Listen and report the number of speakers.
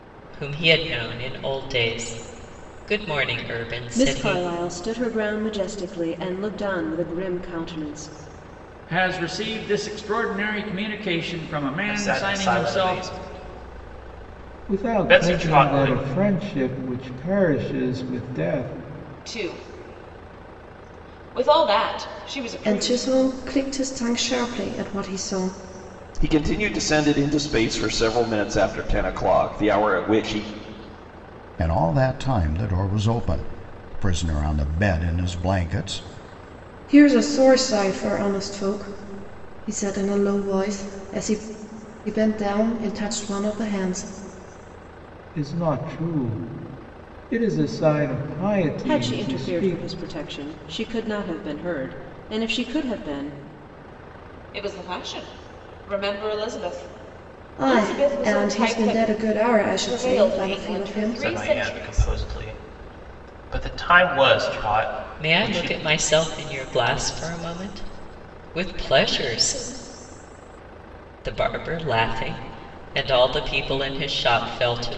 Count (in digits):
9